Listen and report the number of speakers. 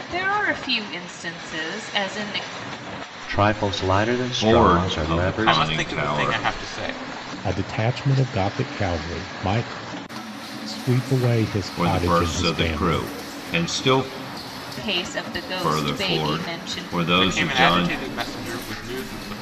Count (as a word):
five